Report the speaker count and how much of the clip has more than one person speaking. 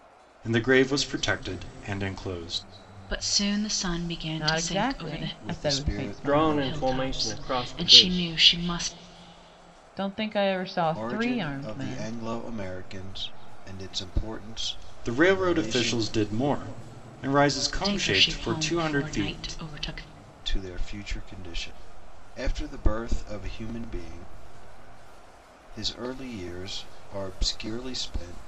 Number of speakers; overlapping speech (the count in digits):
5, about 28%